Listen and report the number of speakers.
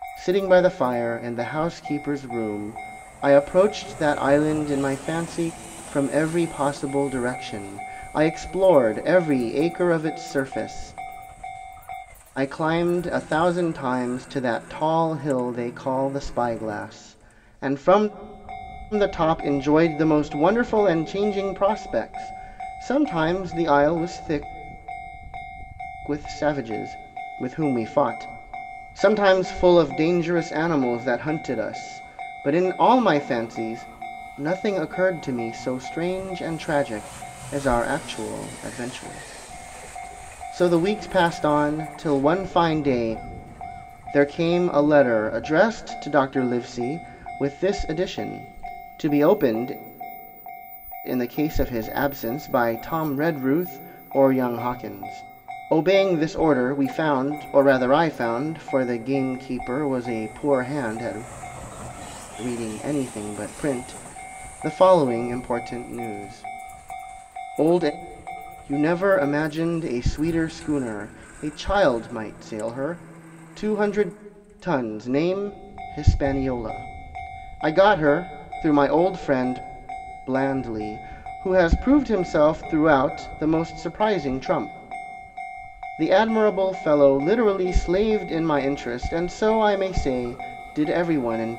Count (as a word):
one